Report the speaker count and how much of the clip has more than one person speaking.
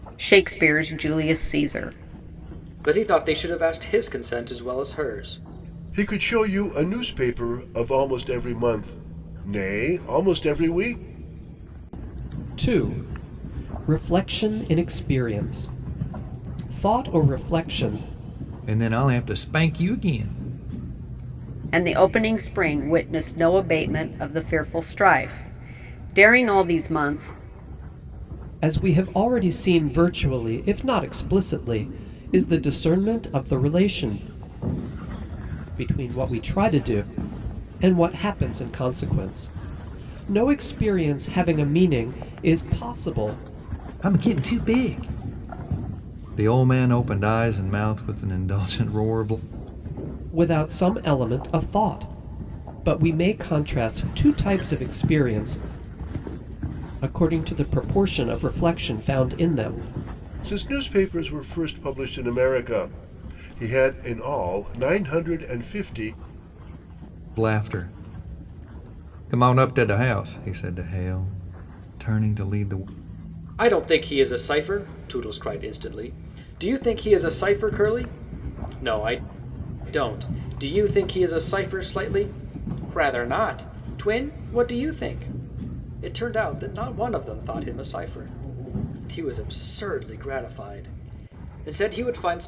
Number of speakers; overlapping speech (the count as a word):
five, no overlap